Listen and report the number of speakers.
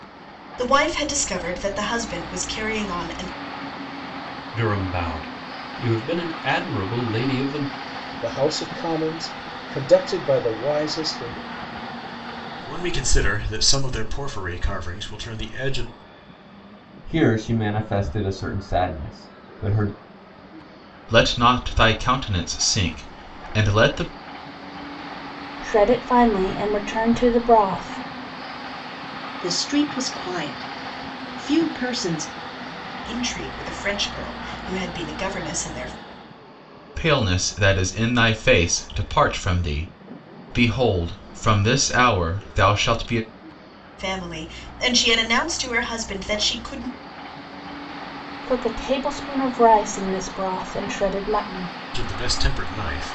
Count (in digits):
8